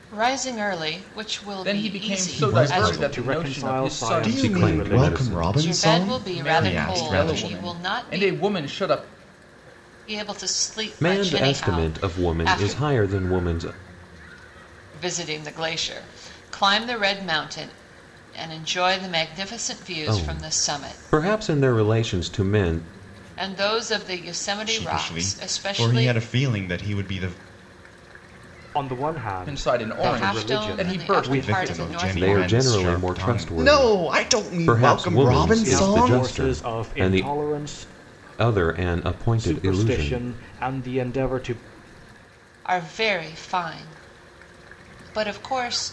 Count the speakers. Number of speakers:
5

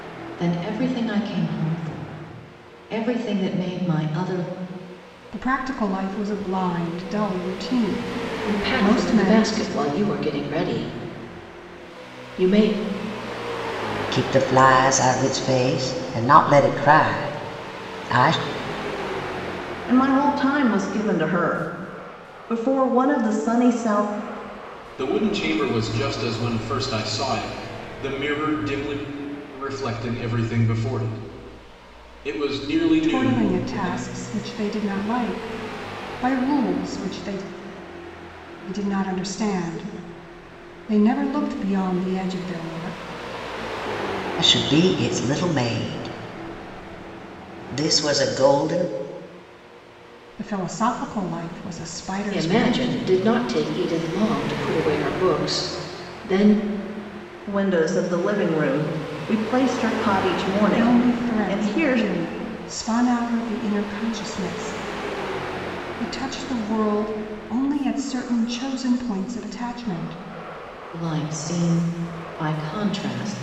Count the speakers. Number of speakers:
6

